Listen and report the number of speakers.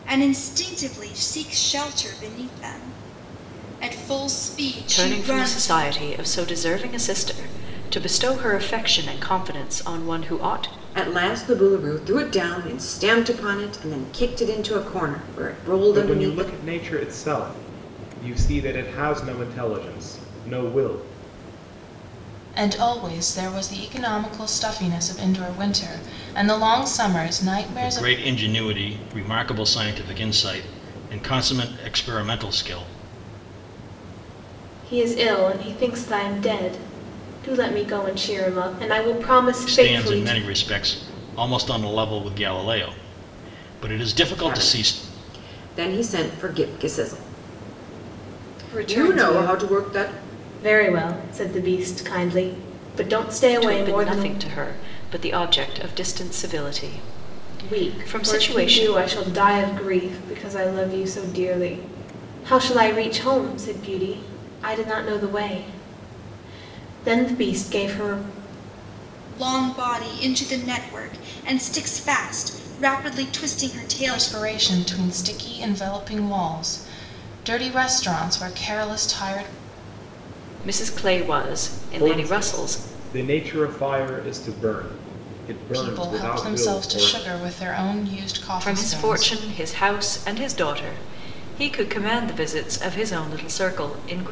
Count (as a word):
seven